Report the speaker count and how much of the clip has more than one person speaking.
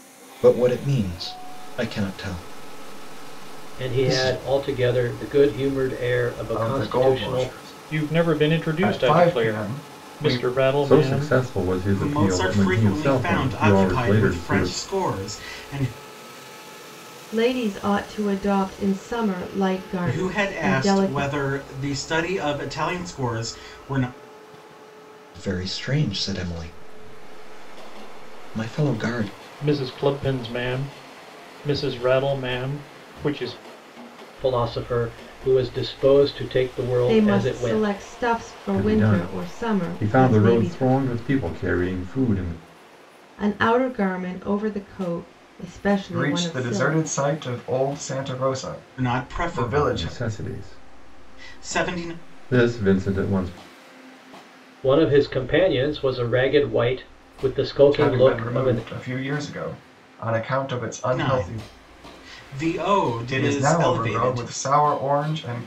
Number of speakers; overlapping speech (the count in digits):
7, about 29%